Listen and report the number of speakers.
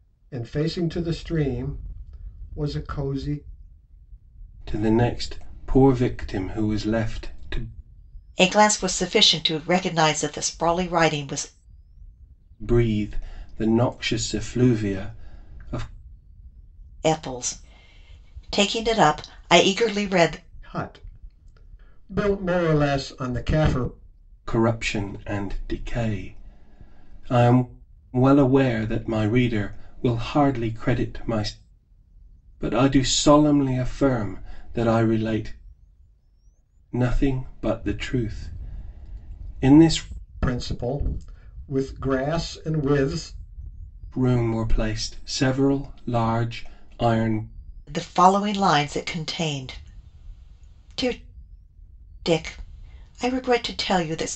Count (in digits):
3